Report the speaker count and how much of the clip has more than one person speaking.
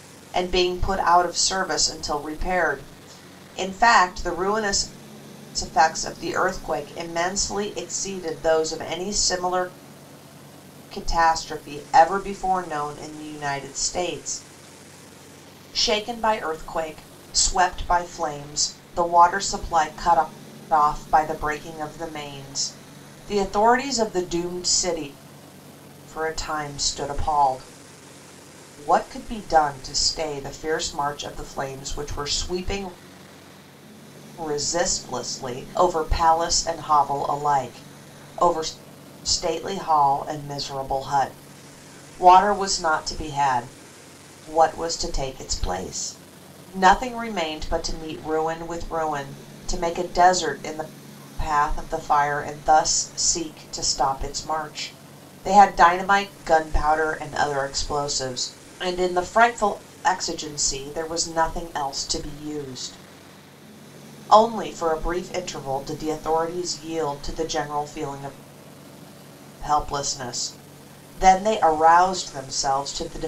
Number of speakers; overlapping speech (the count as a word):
one, no overlap